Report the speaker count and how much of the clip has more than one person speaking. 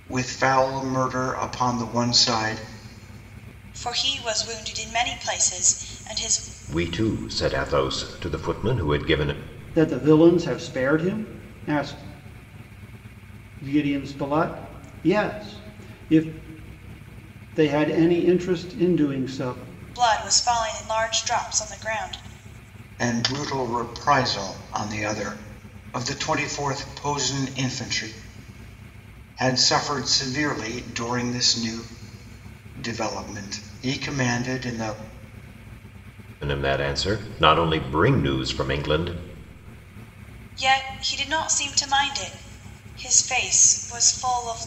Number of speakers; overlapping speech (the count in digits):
4, no overlap